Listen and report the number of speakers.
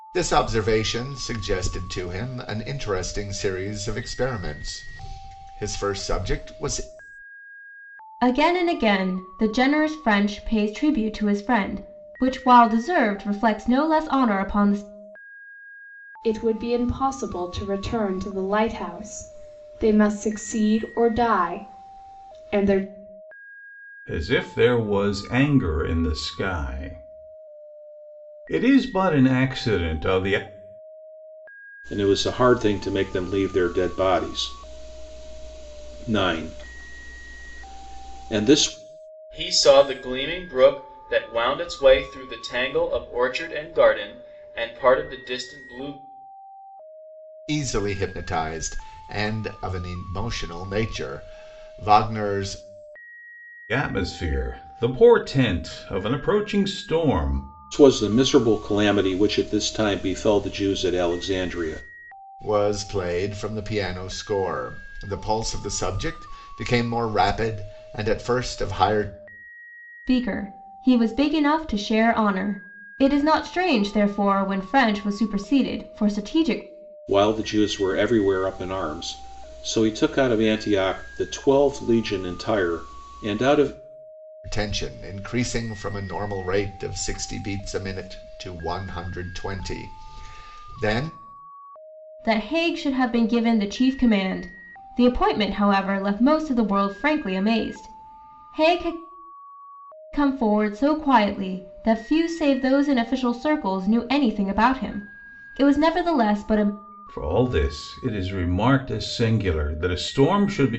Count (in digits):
6